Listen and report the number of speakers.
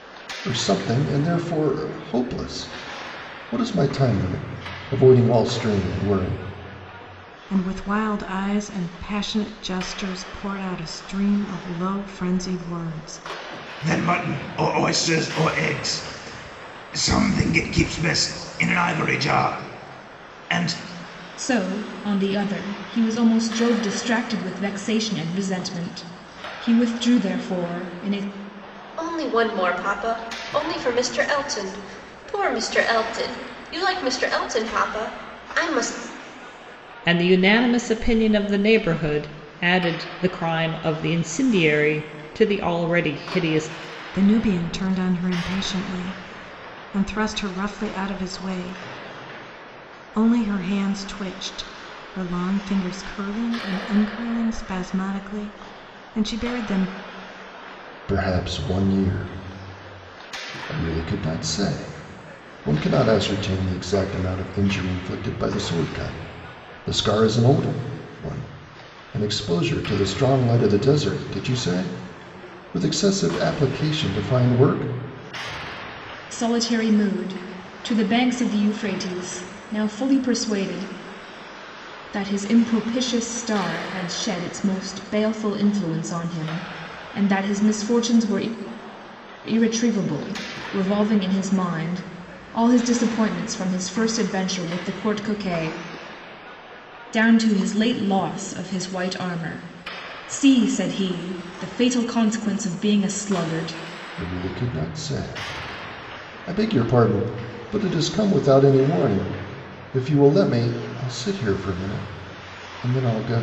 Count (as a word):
six